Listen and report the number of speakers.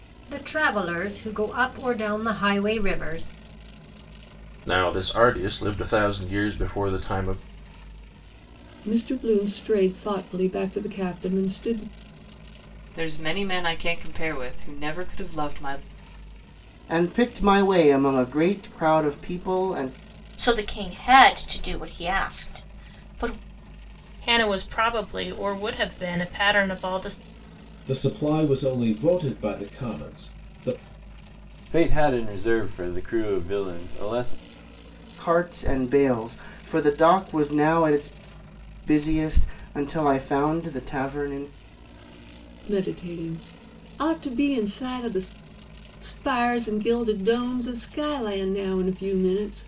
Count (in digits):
9